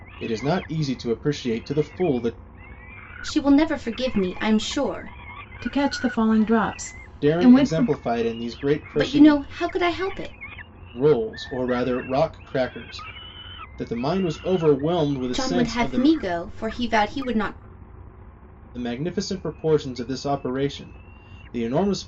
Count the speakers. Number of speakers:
three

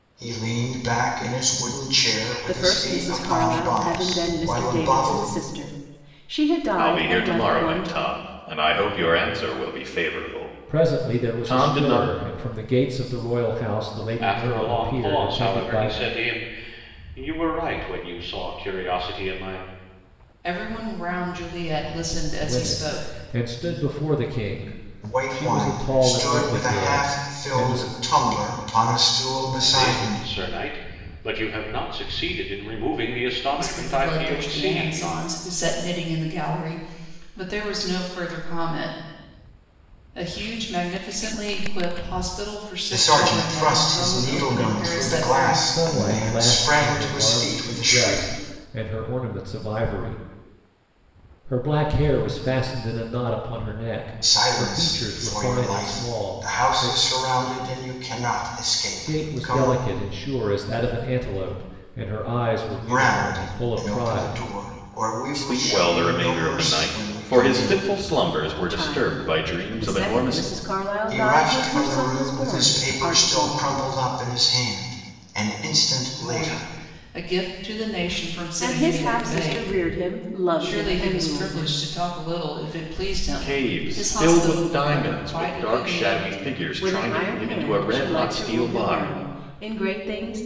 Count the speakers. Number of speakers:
six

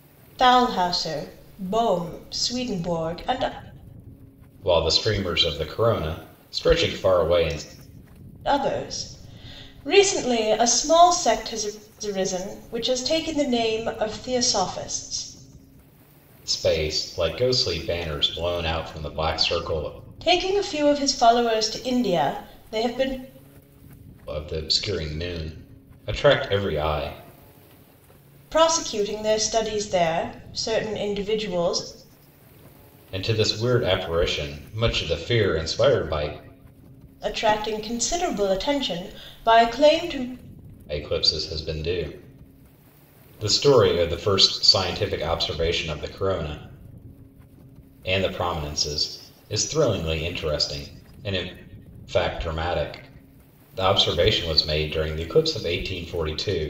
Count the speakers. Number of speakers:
two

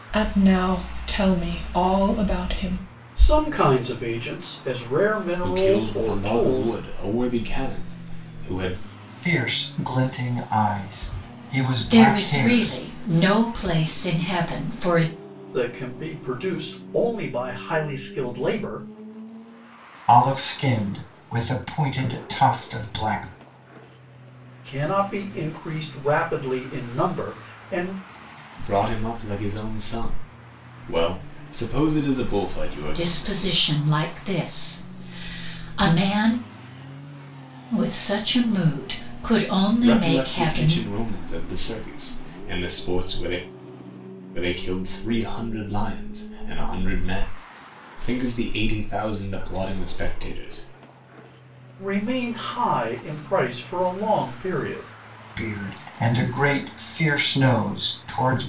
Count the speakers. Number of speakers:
five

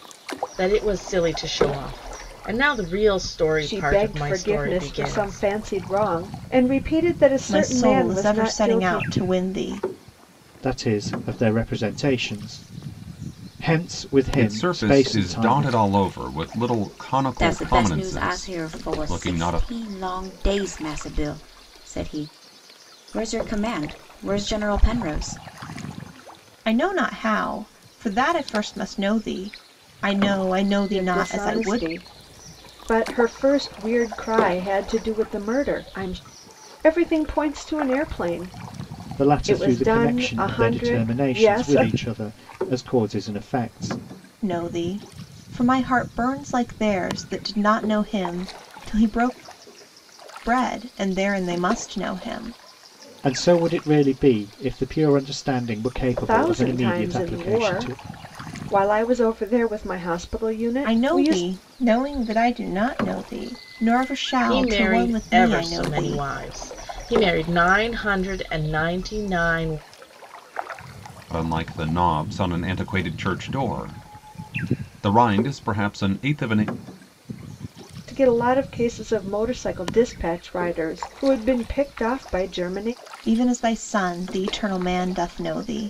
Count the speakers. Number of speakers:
six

